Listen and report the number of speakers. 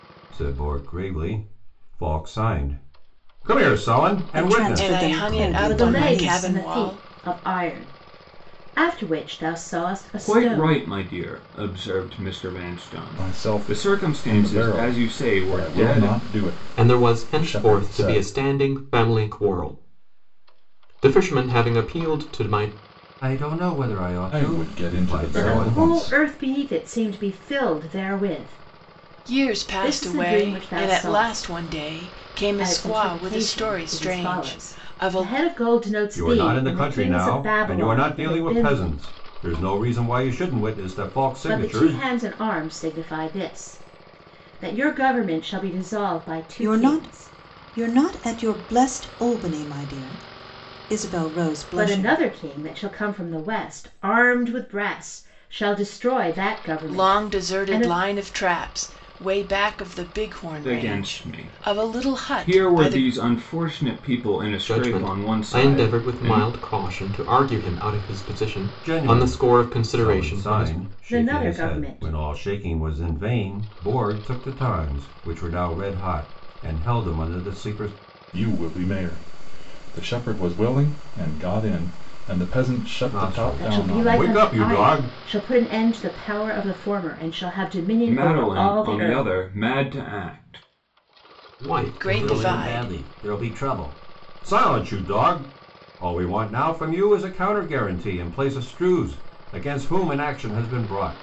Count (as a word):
seven